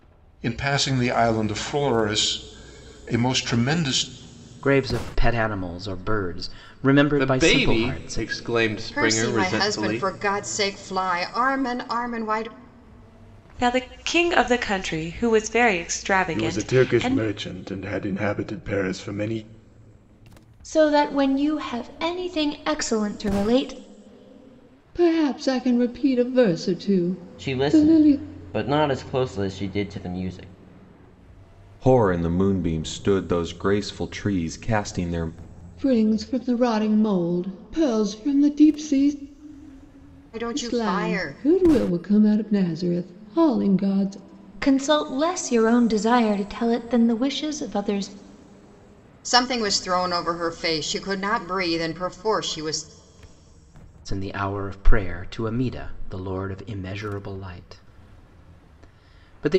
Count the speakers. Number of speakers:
10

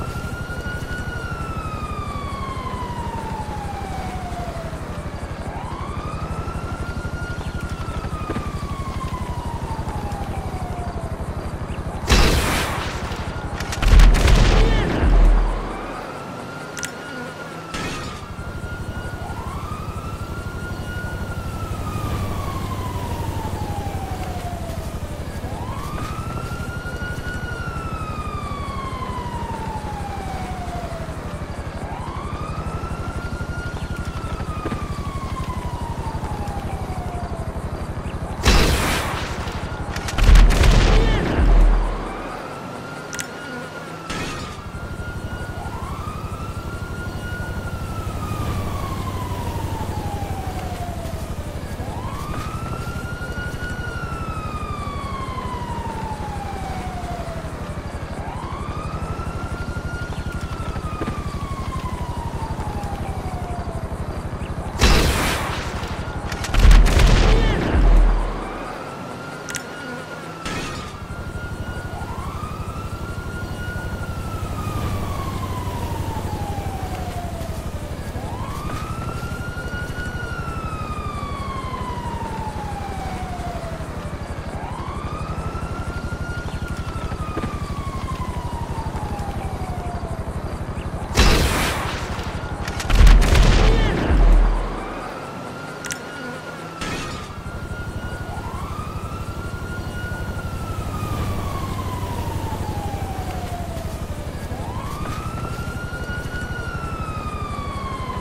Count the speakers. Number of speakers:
0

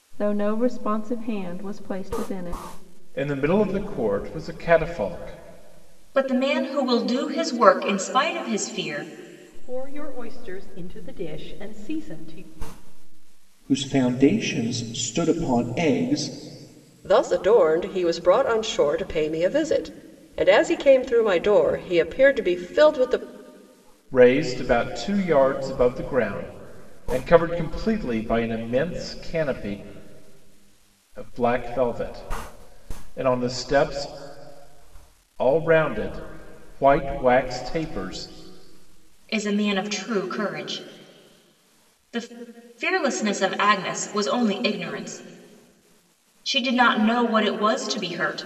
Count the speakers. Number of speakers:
6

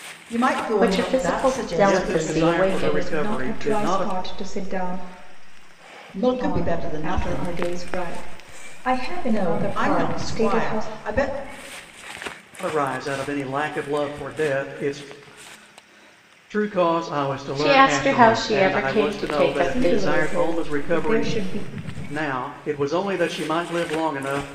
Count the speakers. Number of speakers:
4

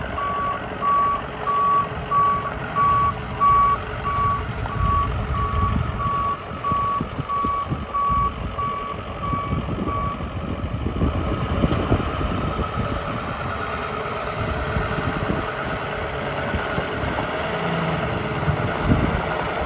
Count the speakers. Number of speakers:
0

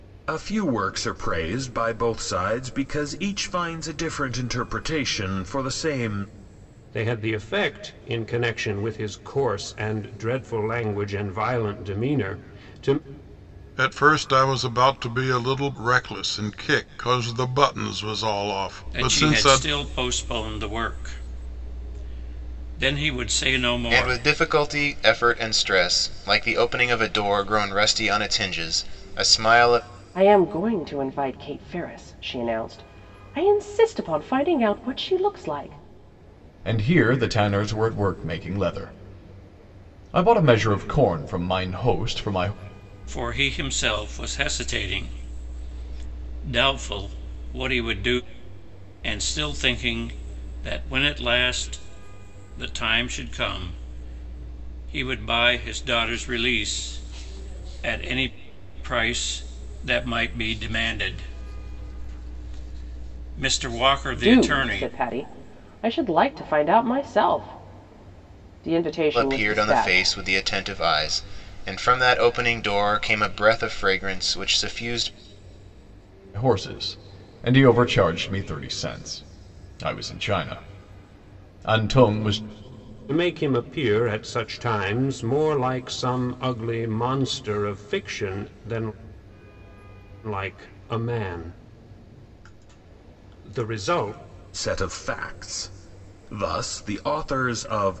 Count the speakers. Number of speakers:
7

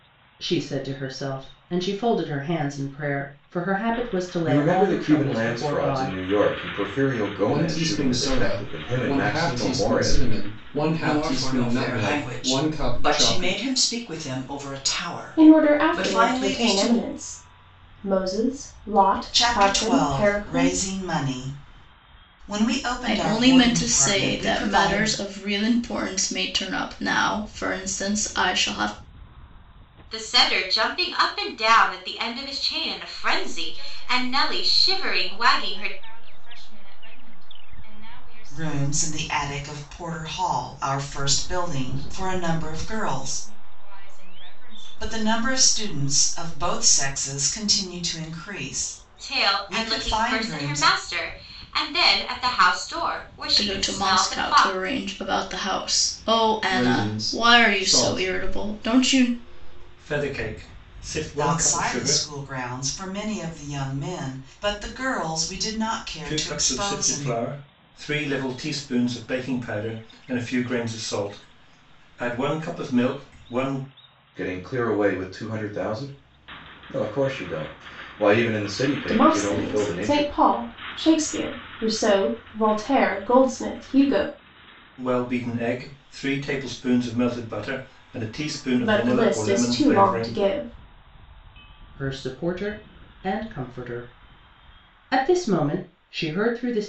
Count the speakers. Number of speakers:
9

